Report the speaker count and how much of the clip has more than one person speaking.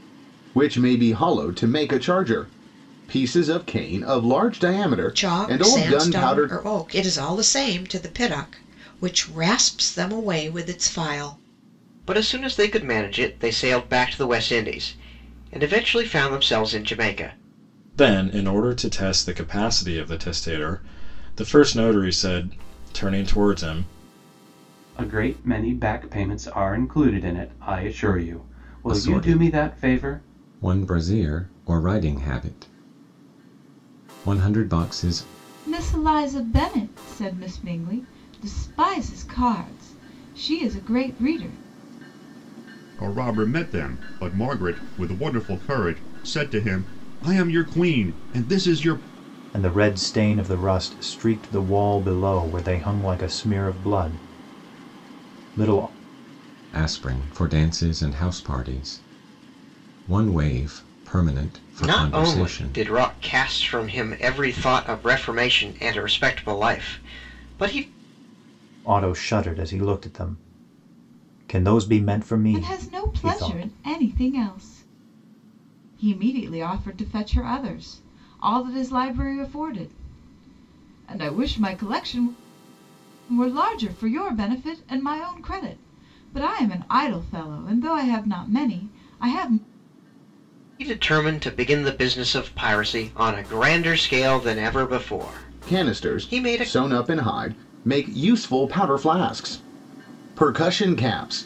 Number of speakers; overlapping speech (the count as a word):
nine, about 6%